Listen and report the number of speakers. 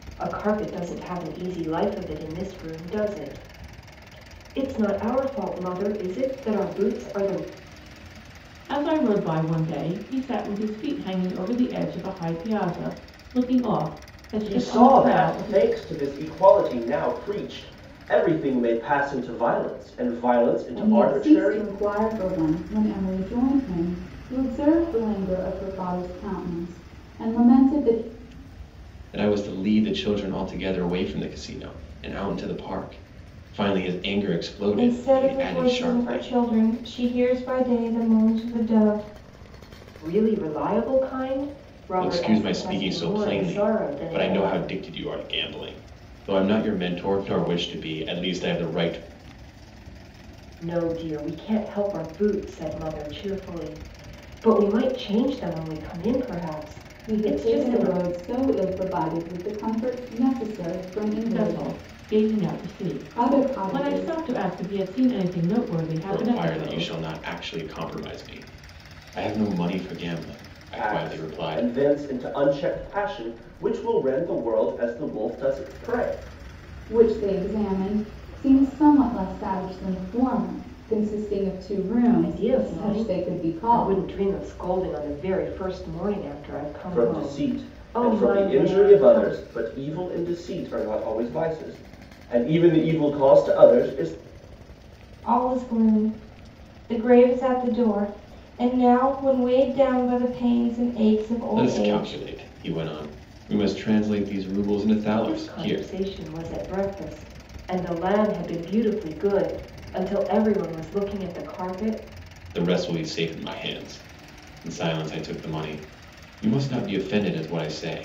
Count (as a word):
six